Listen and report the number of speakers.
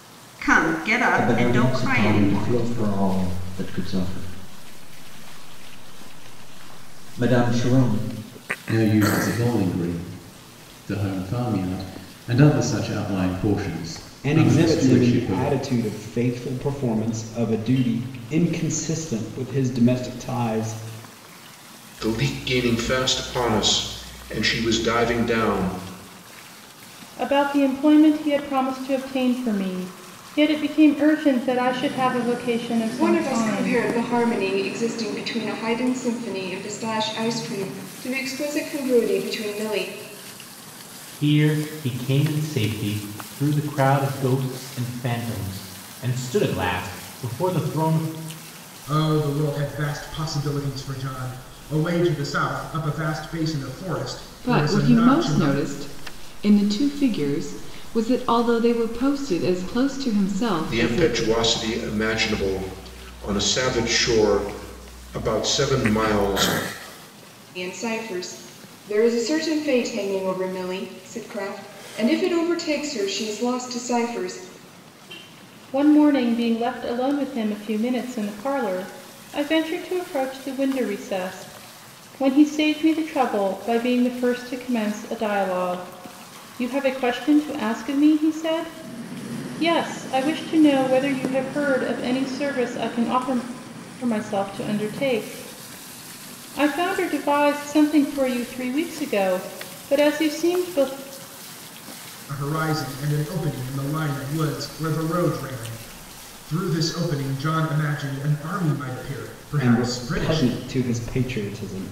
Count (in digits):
10